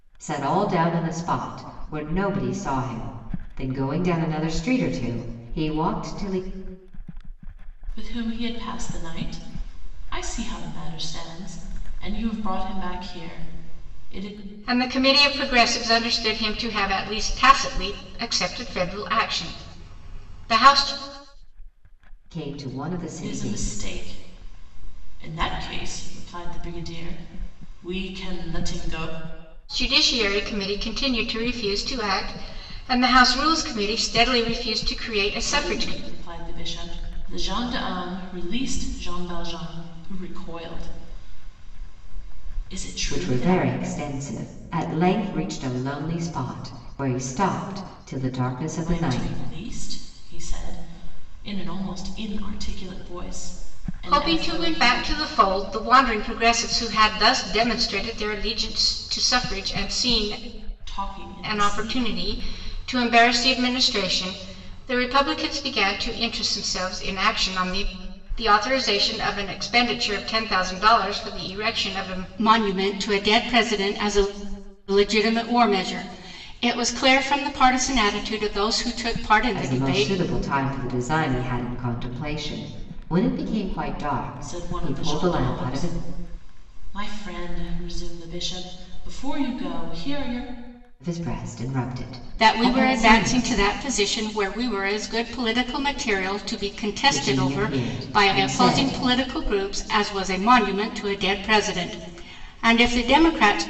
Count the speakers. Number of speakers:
3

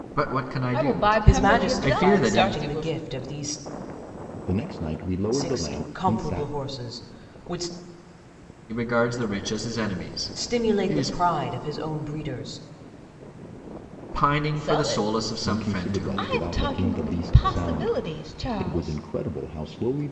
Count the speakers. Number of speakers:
4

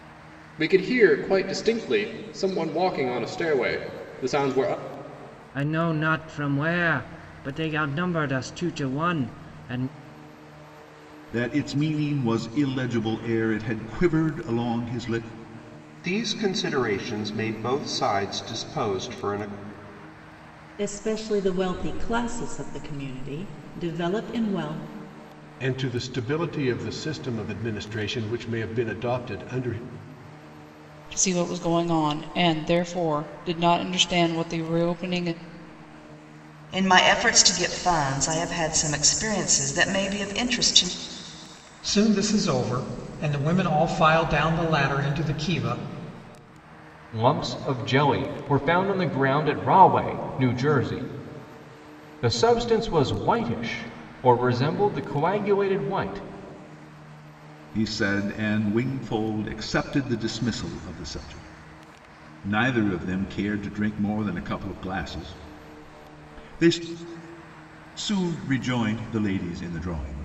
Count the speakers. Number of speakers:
10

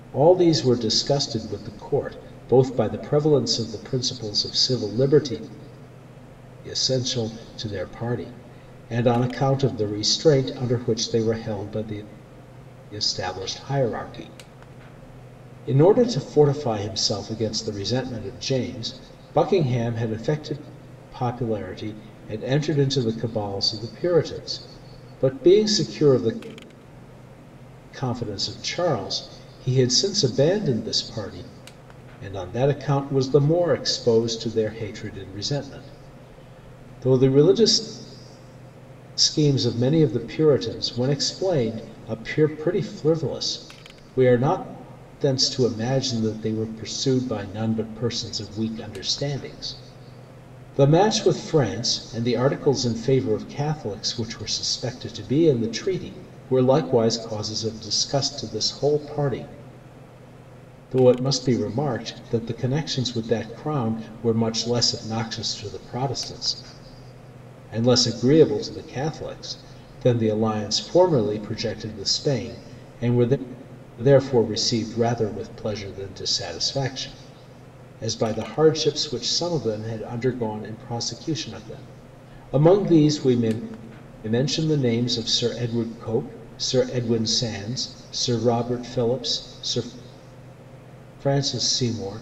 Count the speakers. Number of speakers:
1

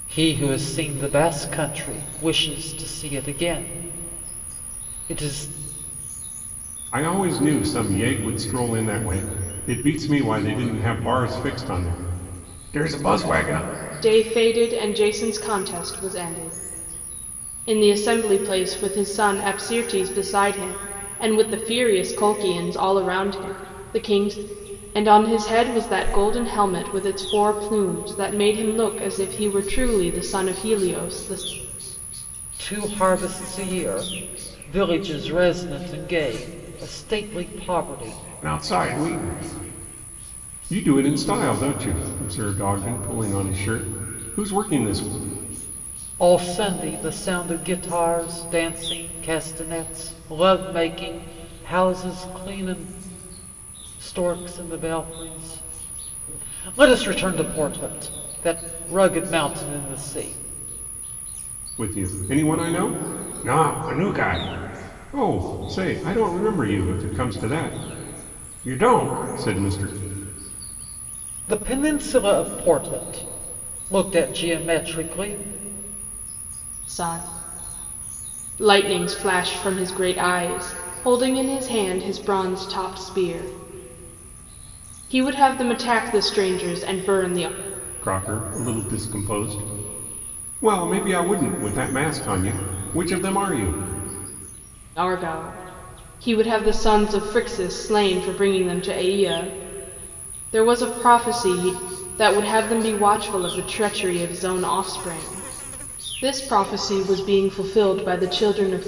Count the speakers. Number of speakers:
3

